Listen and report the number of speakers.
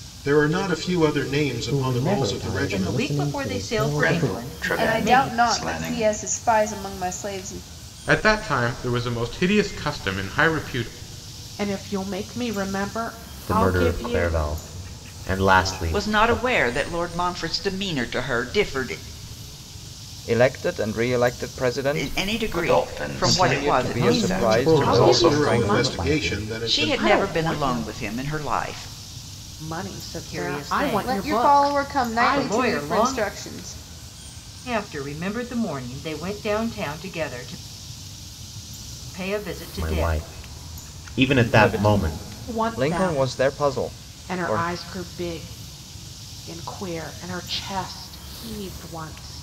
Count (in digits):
10